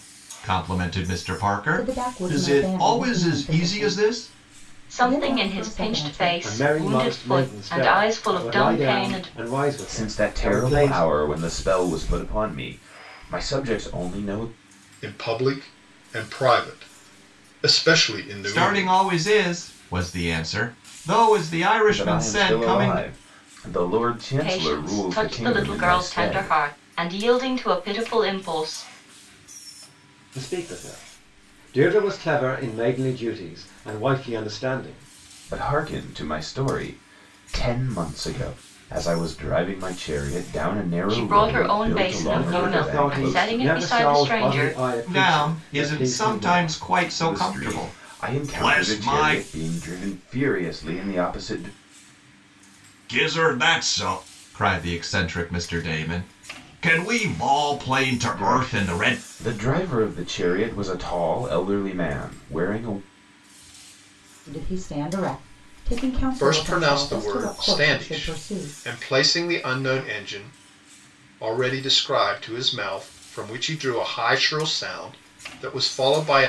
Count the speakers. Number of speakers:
6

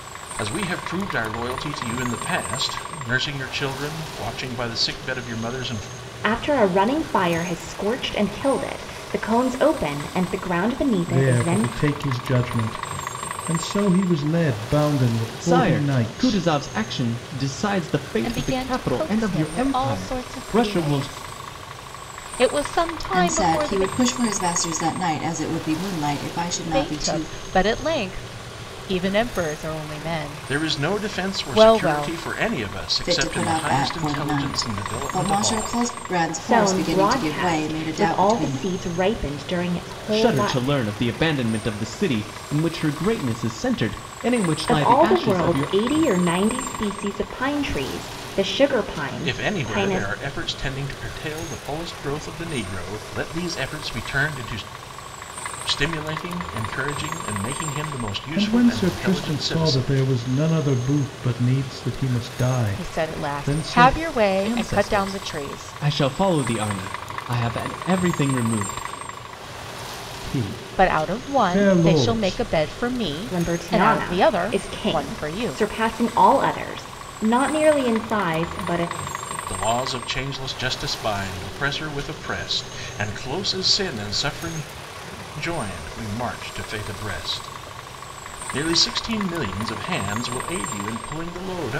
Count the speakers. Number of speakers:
6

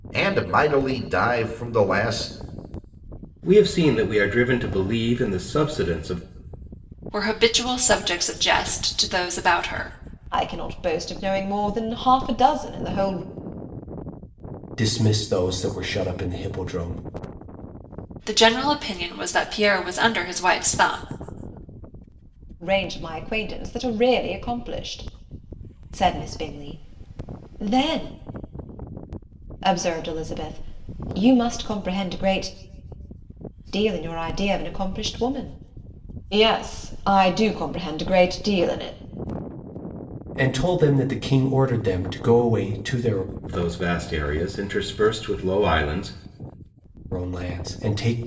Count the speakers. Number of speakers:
5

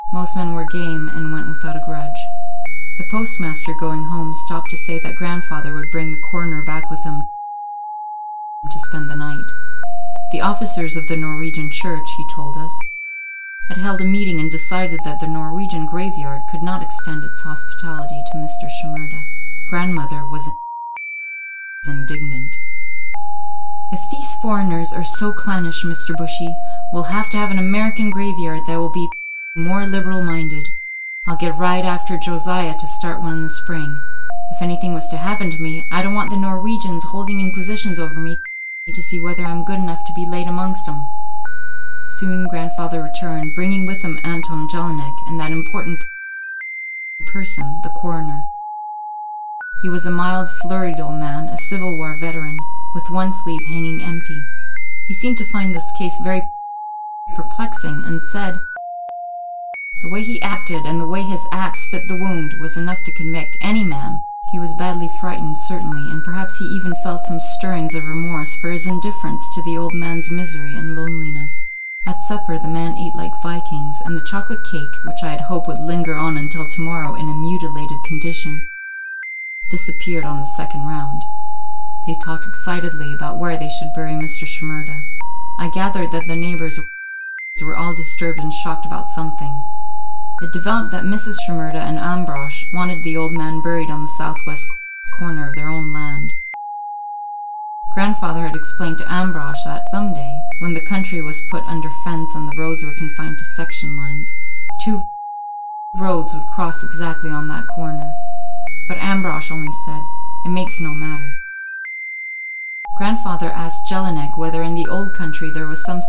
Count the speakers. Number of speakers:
1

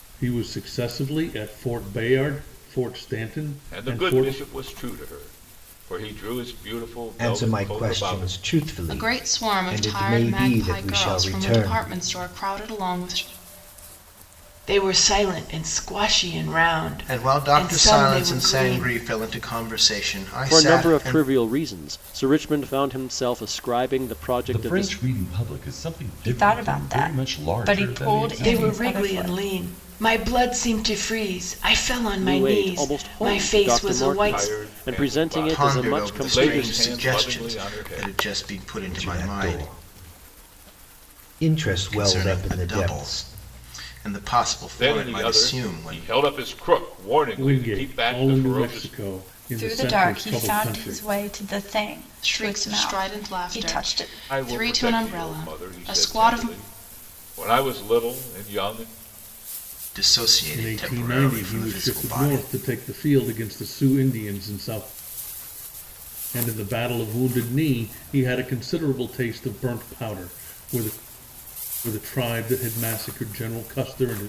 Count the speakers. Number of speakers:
9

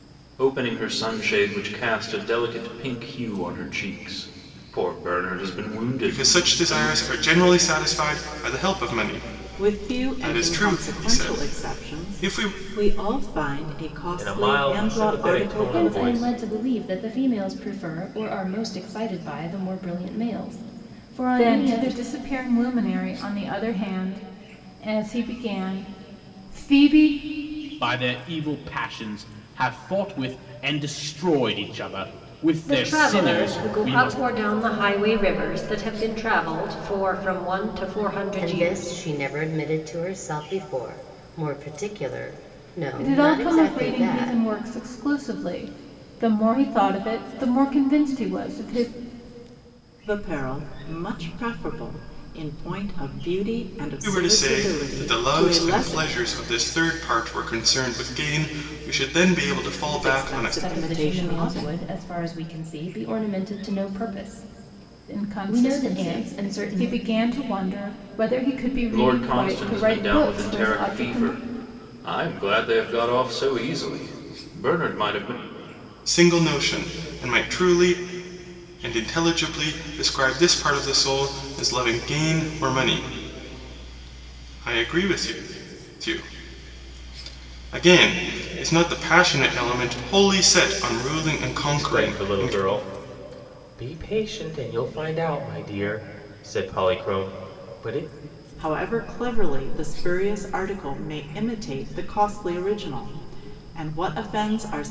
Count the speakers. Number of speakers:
9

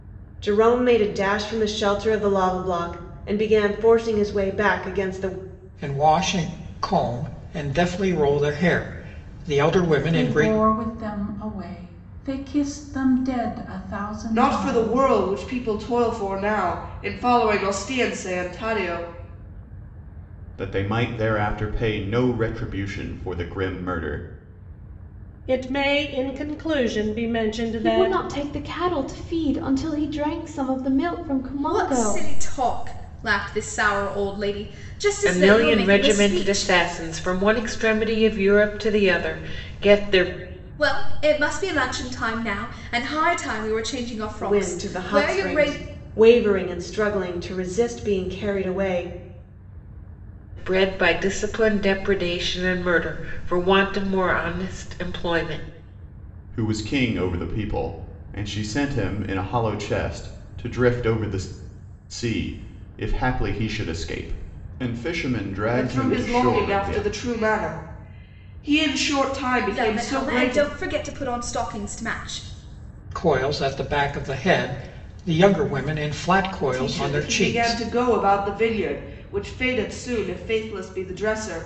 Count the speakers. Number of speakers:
9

